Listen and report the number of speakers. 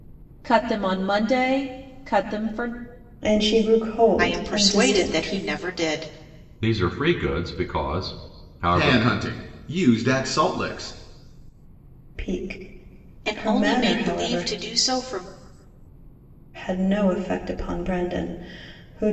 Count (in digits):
5